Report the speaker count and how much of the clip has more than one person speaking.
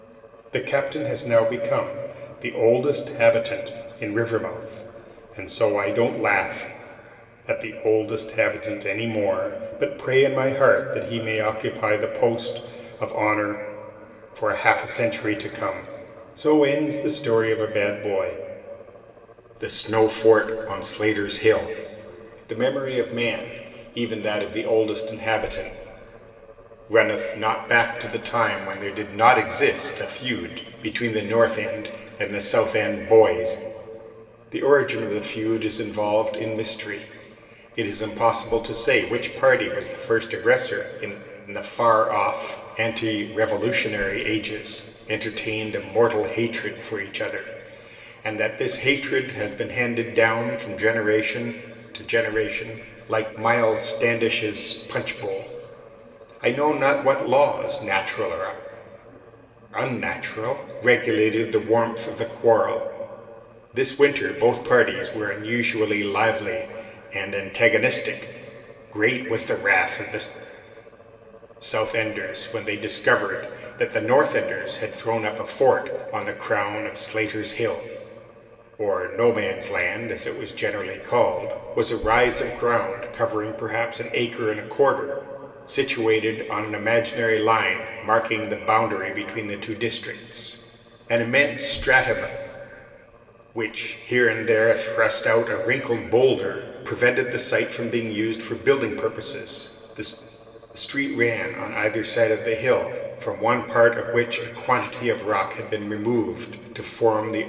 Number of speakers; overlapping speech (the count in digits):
1, no overlap